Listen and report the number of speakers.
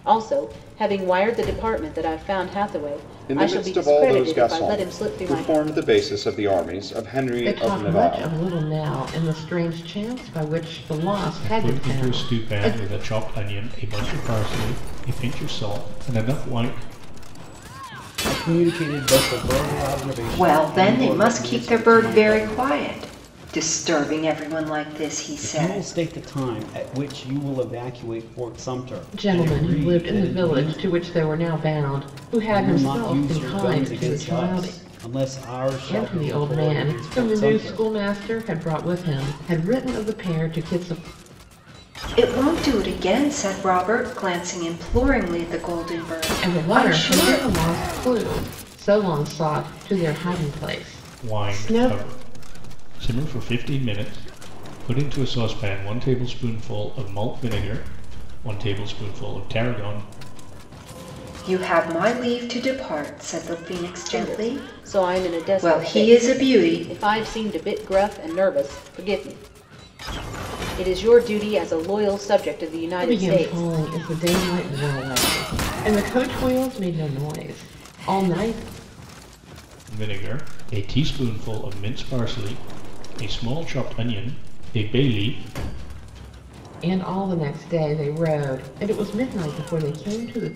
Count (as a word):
six